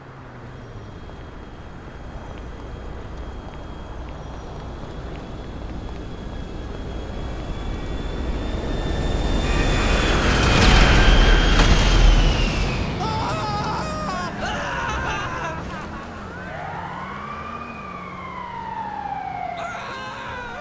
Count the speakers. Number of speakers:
0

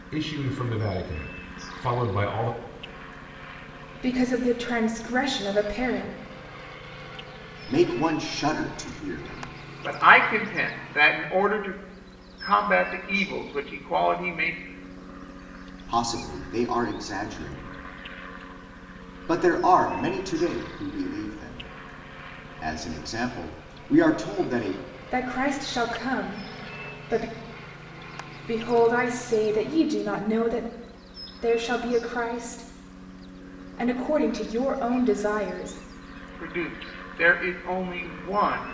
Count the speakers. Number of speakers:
4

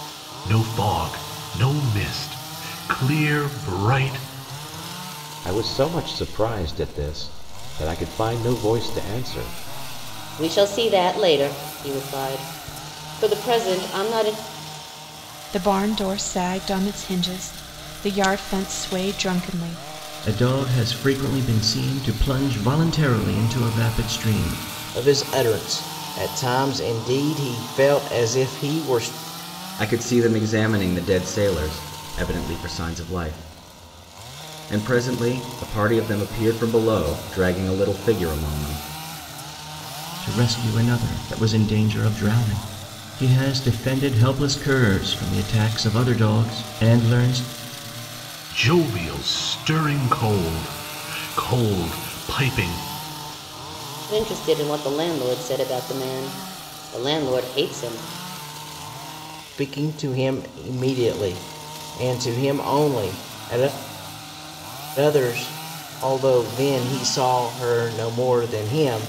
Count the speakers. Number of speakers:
7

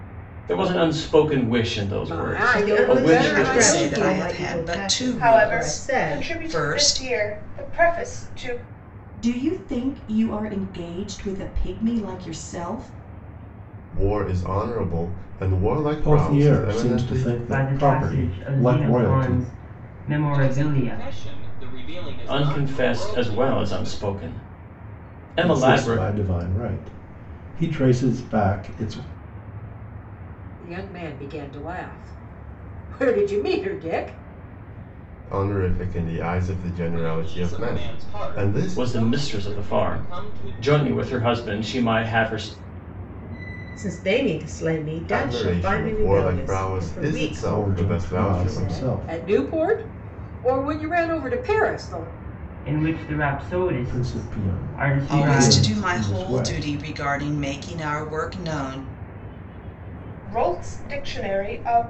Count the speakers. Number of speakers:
10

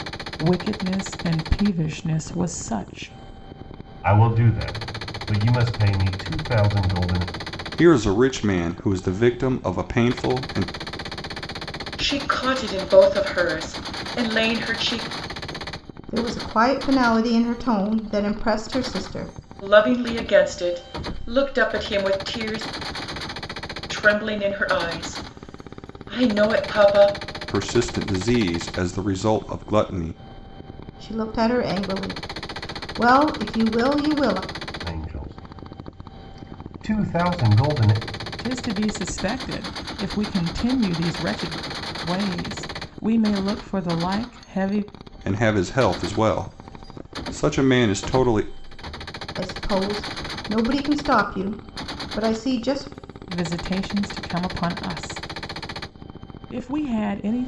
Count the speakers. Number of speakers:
5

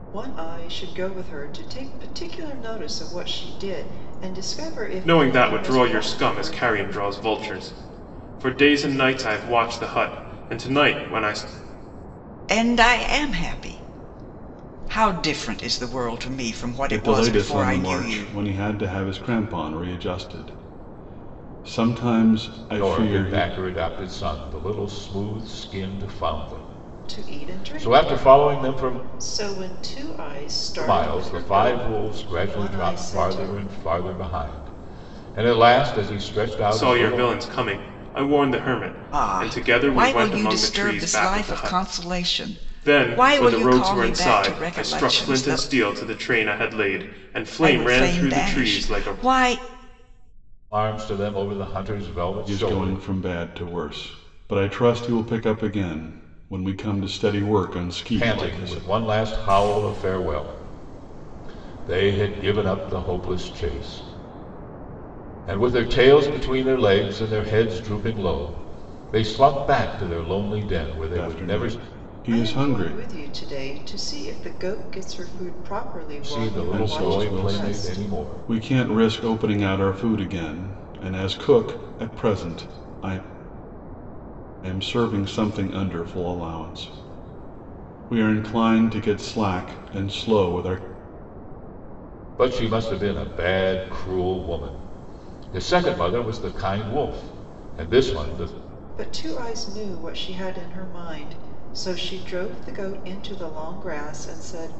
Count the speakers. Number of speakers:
5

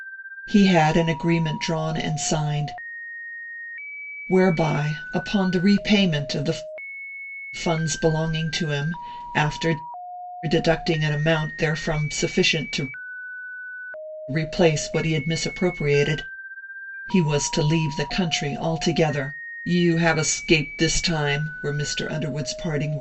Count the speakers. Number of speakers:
1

